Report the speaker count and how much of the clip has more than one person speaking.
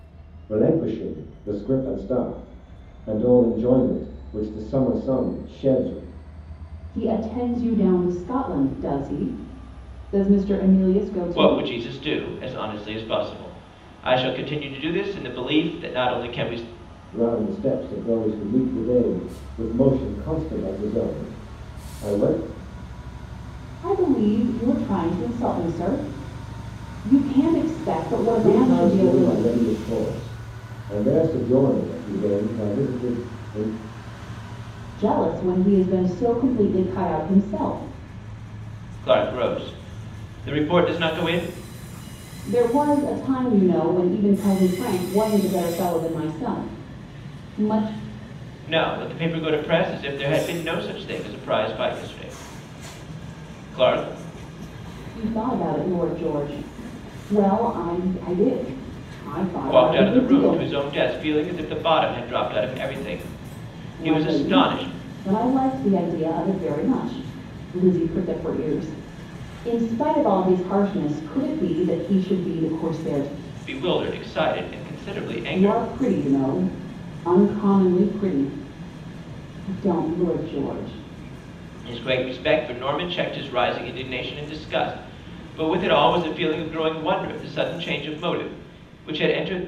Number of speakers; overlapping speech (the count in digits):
3, about 4%